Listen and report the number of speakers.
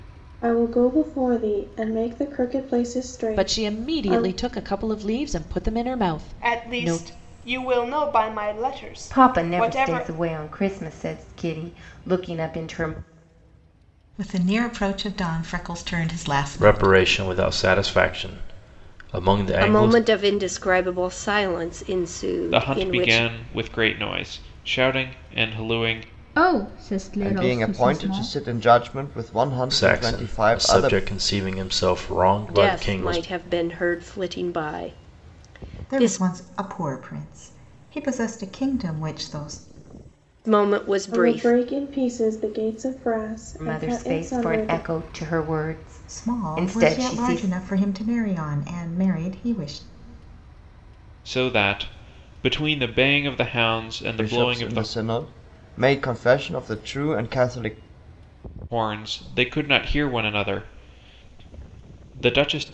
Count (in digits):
10